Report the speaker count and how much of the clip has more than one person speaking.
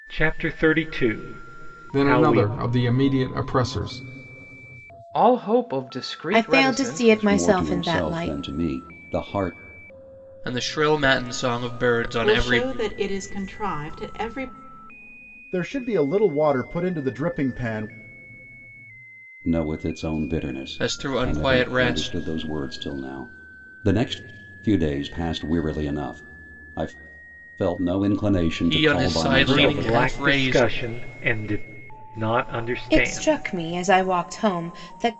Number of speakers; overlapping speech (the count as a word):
eight, about 21%